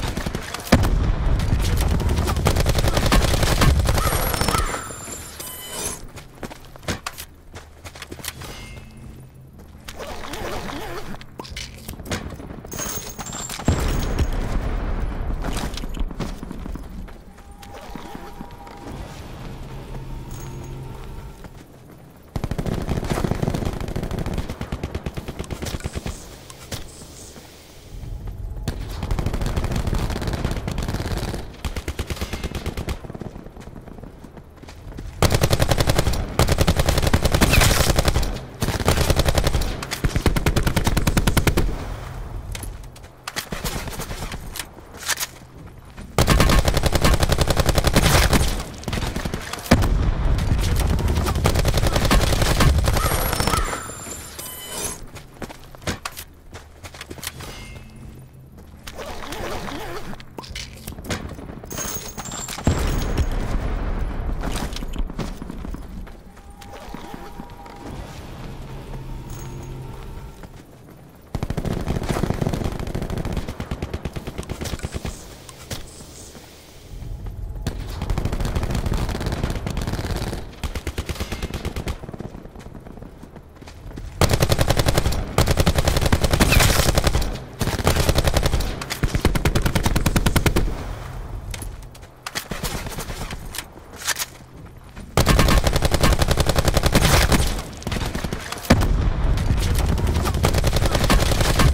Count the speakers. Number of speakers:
0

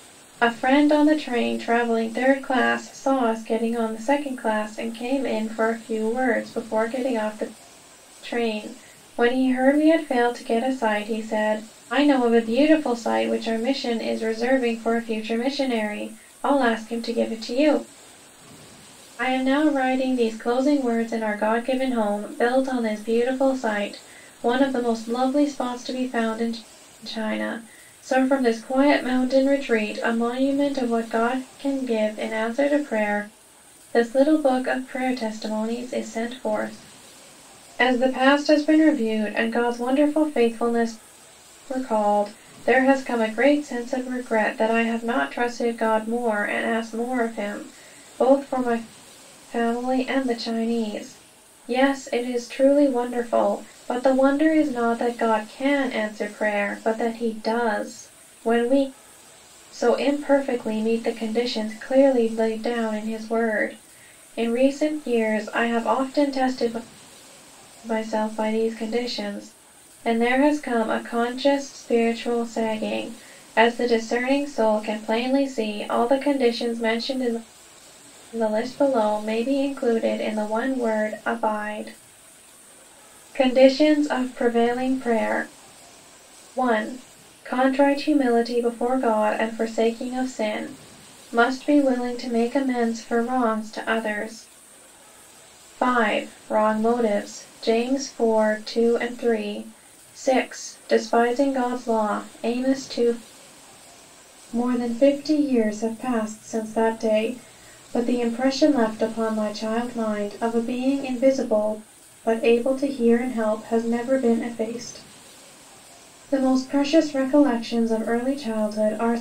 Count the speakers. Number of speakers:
1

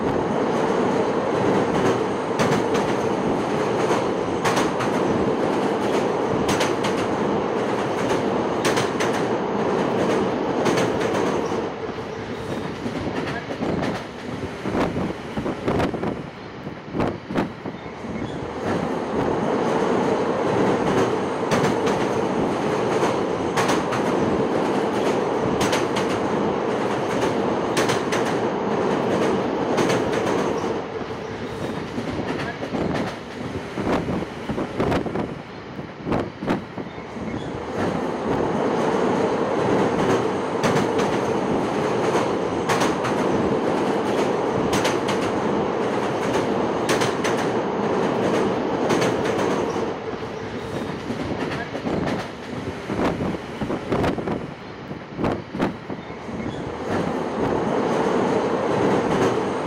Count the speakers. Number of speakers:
0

